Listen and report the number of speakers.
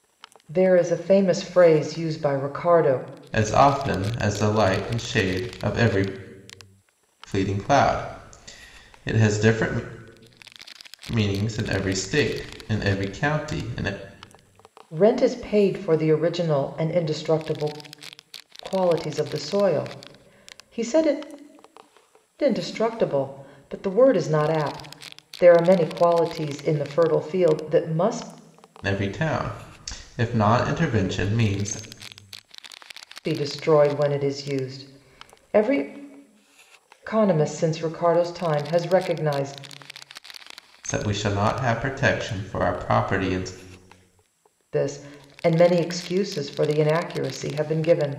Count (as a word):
two